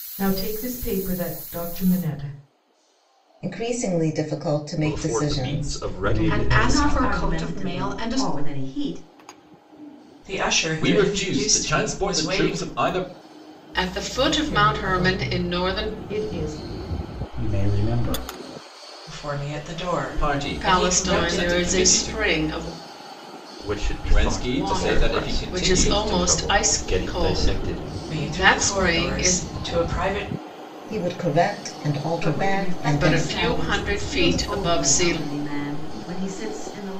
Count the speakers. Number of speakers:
nine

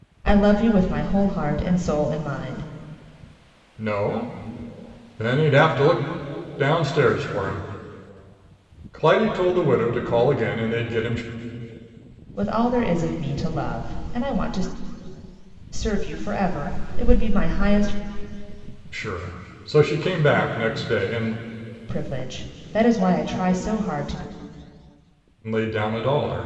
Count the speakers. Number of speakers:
two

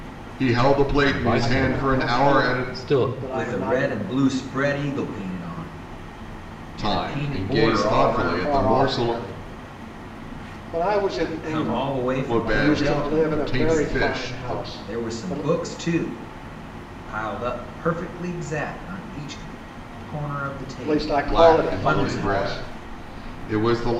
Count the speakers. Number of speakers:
four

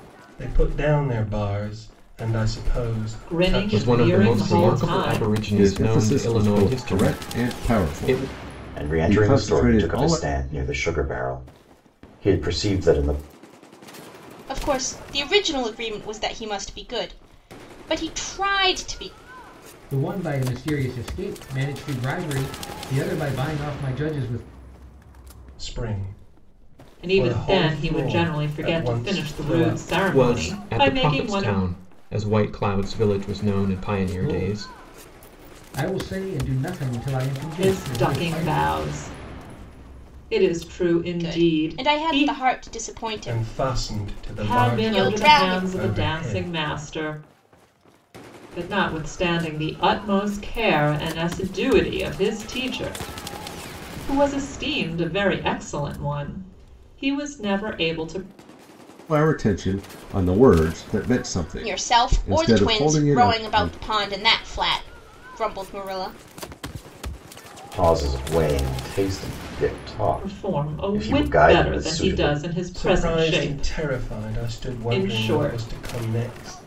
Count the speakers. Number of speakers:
seven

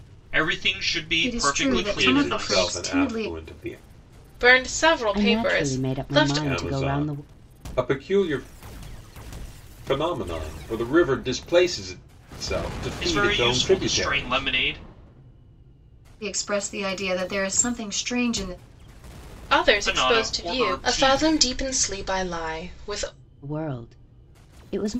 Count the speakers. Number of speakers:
five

